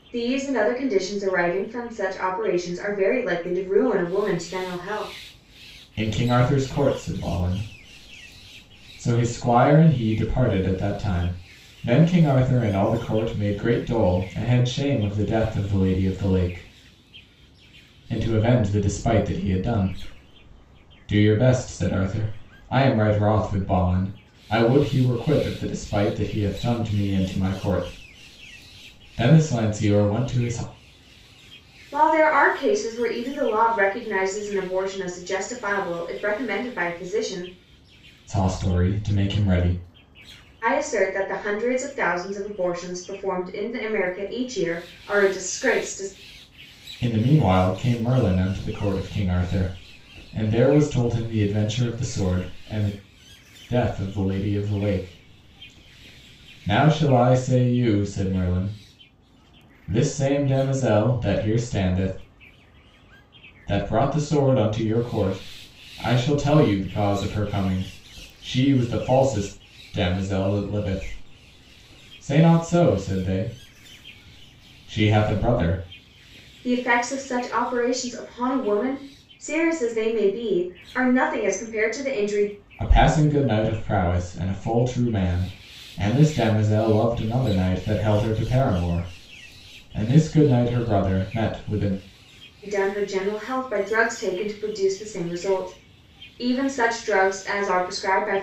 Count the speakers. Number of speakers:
2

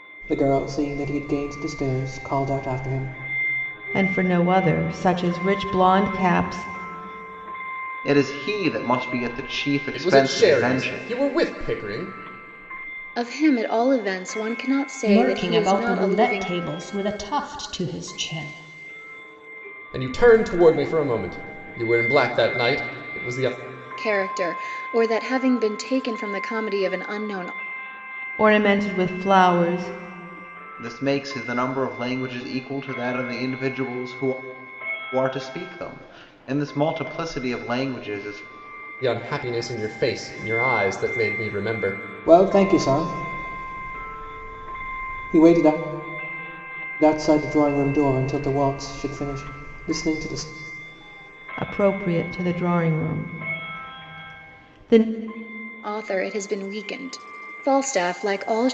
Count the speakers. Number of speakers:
6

